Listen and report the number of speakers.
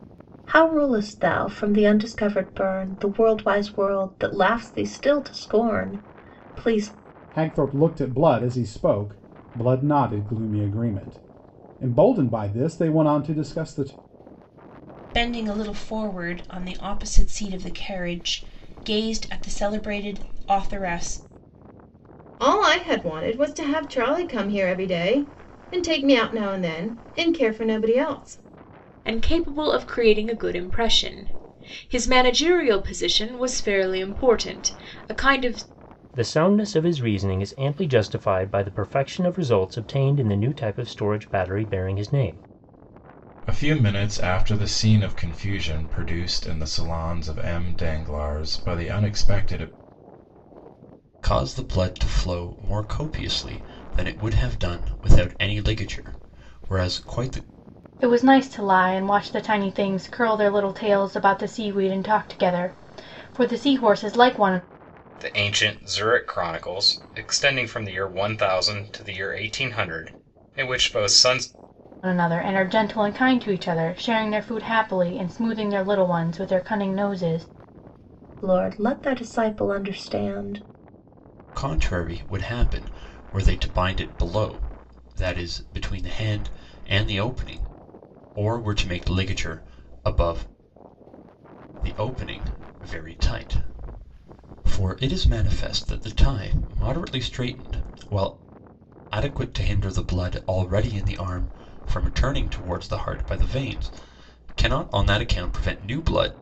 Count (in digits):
10